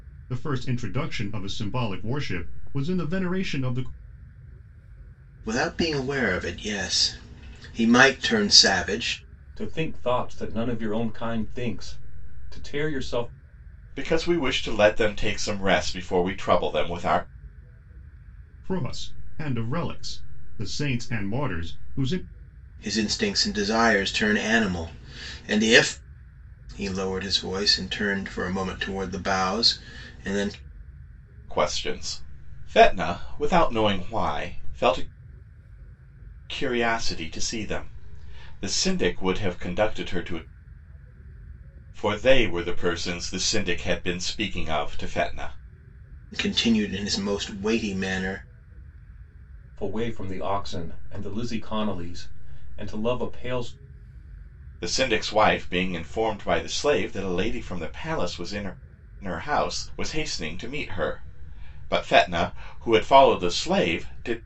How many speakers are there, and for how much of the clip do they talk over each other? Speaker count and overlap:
4, no overlap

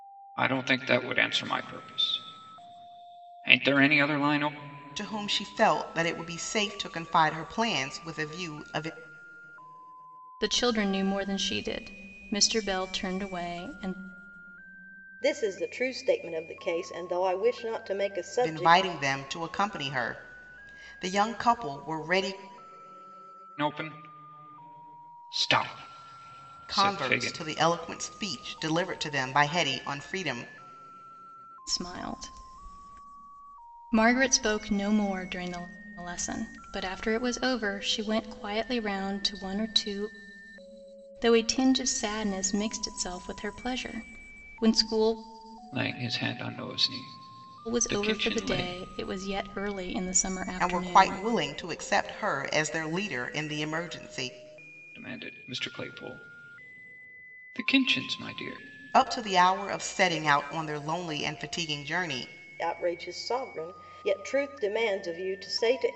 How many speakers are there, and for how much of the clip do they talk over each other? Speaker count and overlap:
4, about 5%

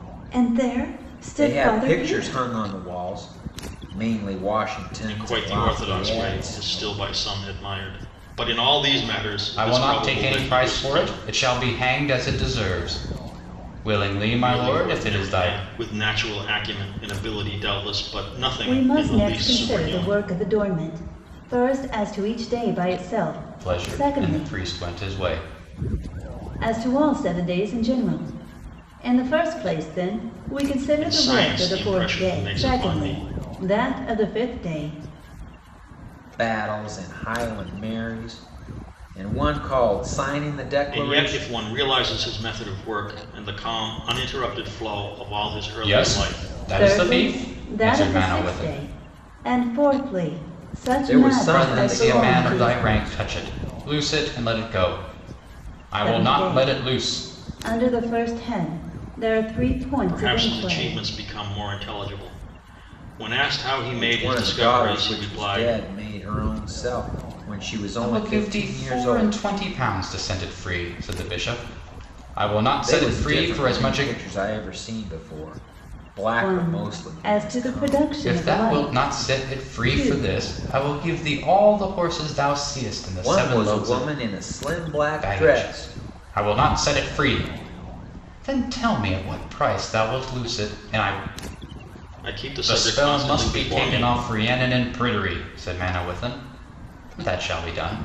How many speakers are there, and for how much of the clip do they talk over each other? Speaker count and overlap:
4, about 31%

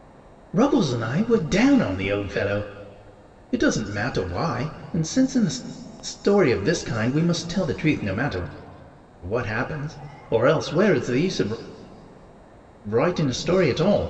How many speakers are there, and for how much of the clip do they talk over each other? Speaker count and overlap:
1, no overlap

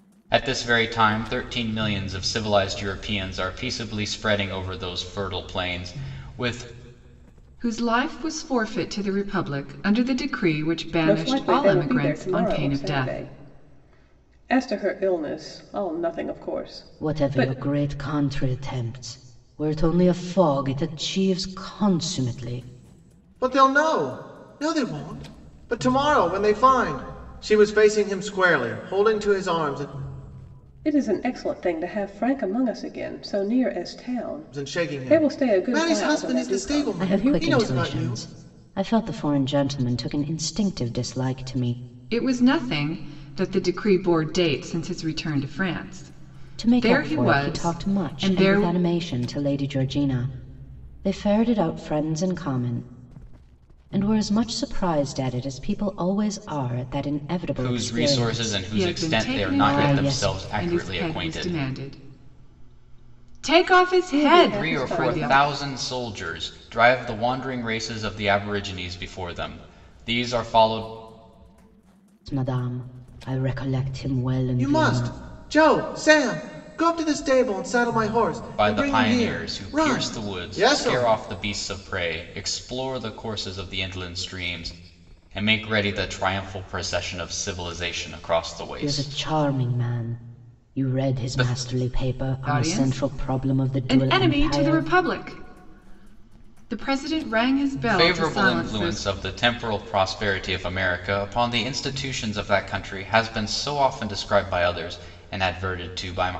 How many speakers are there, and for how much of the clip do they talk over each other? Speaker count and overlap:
5, about 23%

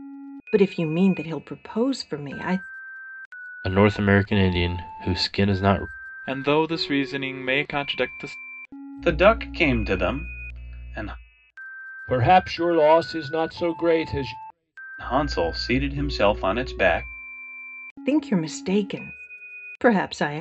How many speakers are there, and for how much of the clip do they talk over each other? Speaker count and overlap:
5, no overlap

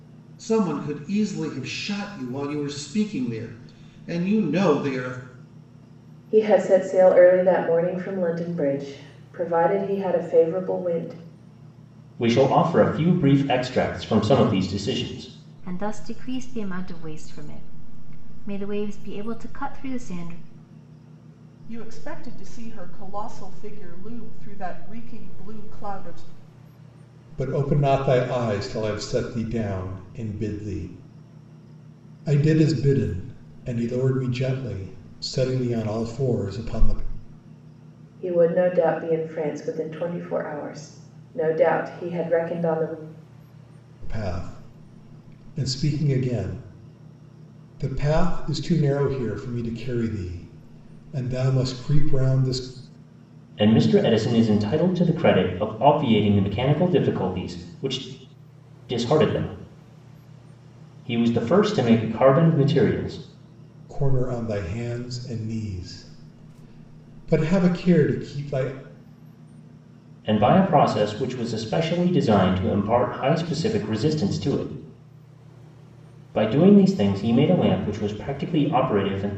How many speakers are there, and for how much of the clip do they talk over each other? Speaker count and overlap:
6, no overlap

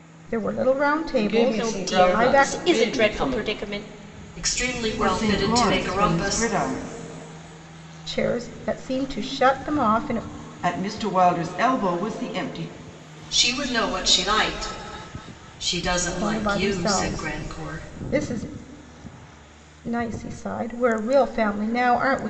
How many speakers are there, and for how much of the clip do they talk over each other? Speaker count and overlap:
5, about 26%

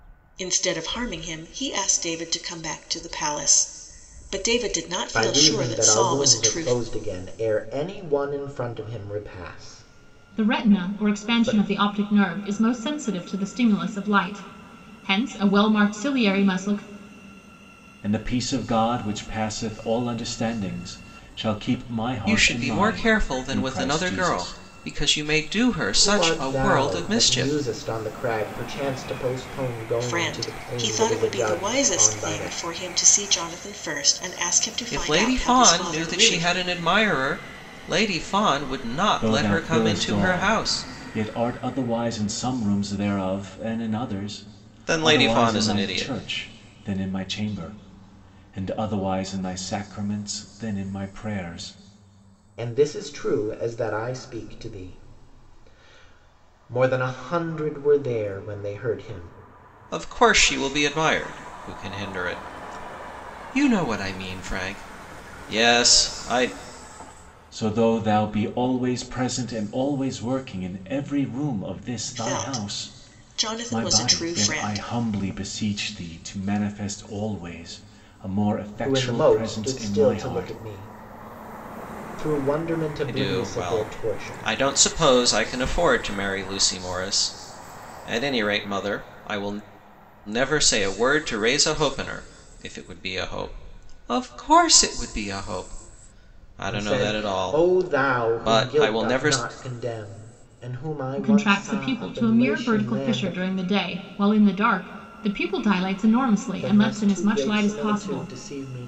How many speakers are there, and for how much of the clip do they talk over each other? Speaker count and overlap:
5, about 25%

